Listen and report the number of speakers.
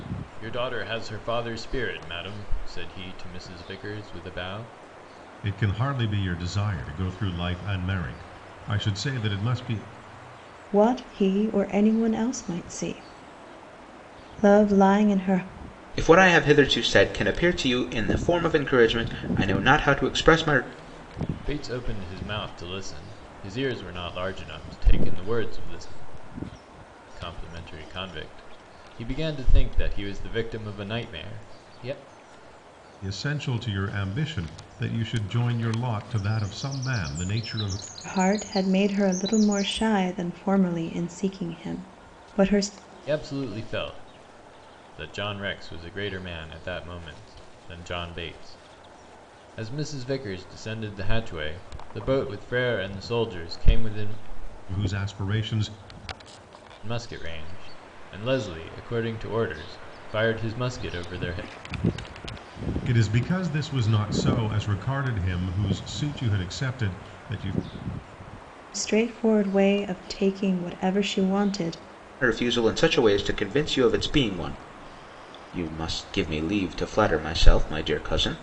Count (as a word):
four